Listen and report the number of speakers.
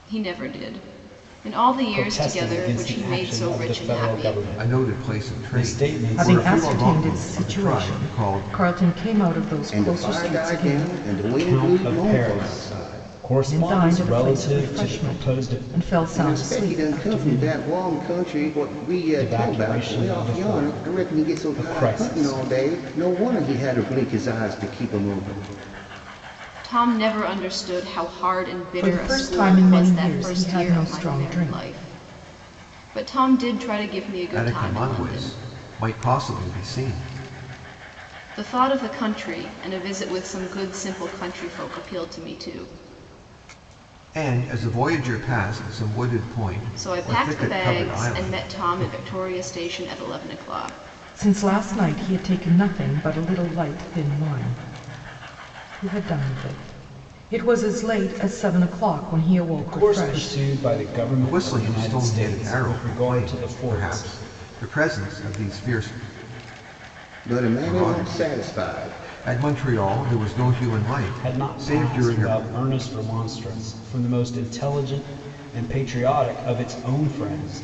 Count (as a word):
five